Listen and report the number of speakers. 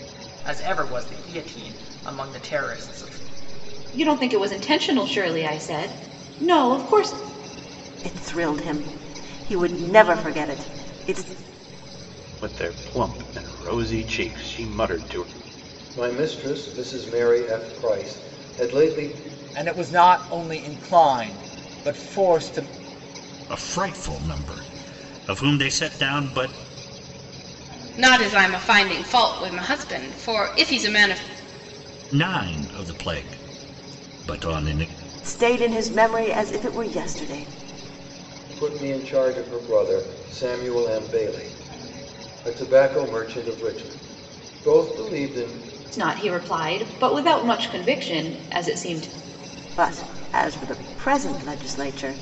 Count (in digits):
8